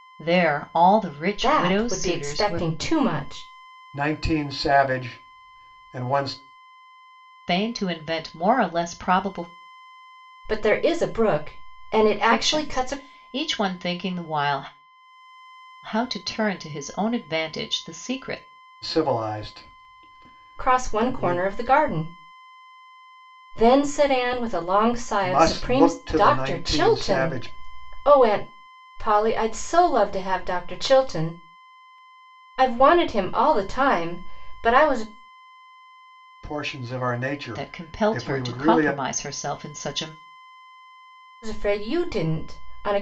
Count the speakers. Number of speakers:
3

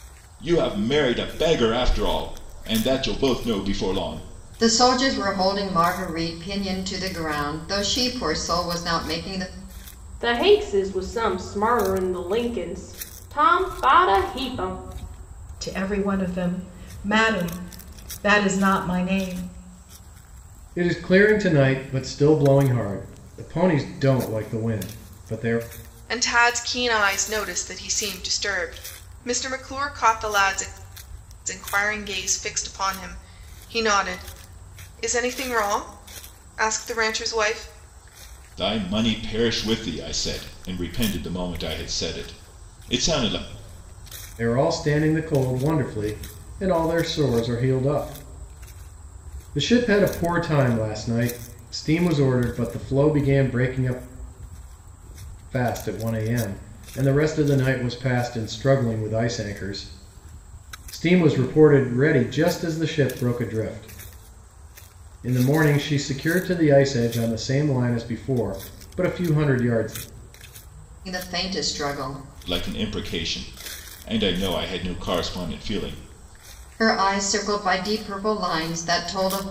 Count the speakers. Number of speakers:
6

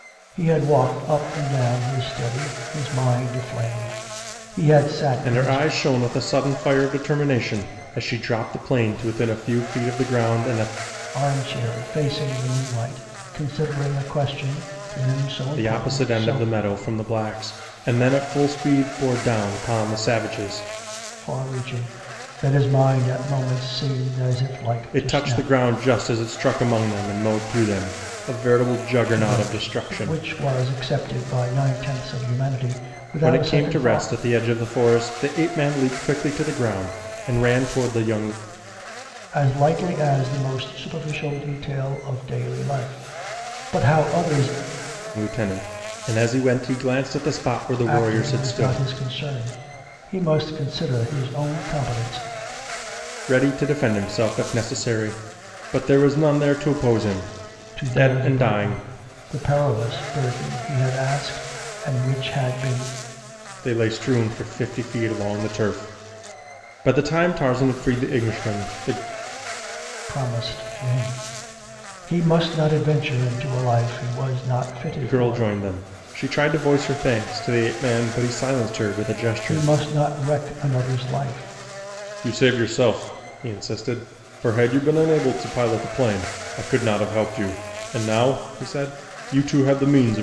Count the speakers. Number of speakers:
2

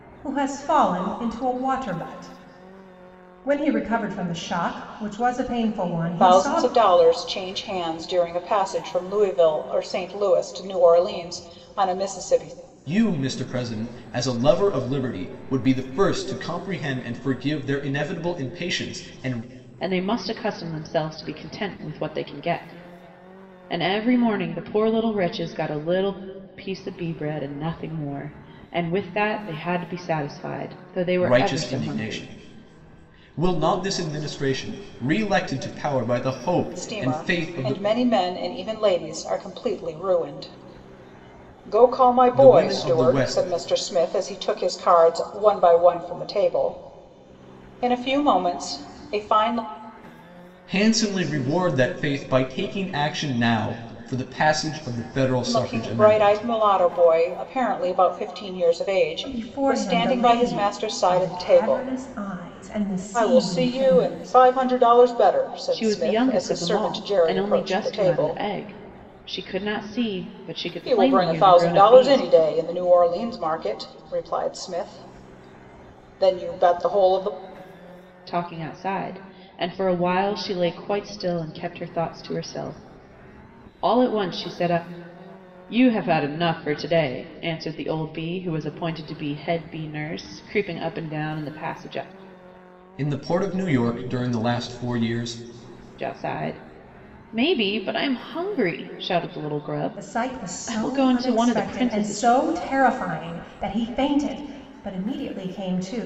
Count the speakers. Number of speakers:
4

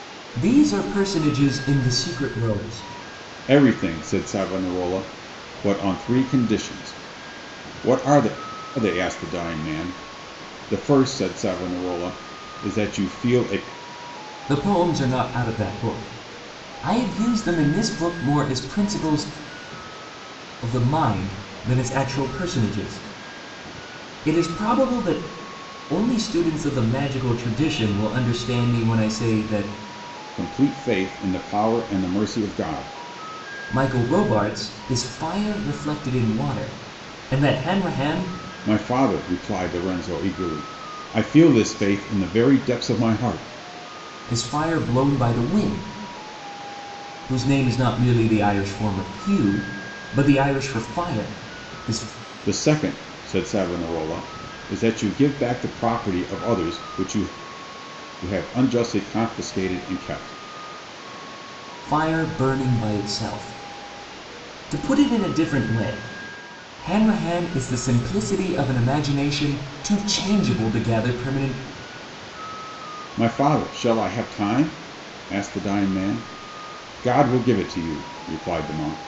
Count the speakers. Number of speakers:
2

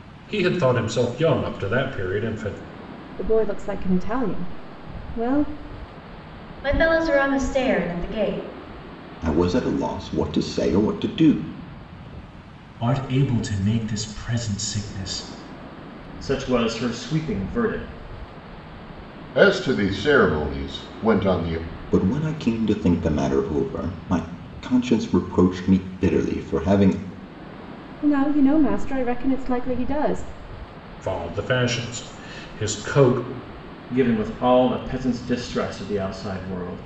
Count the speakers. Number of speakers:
7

